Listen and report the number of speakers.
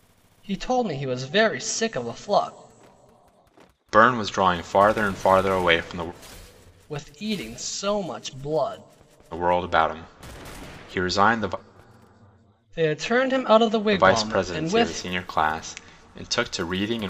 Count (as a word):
two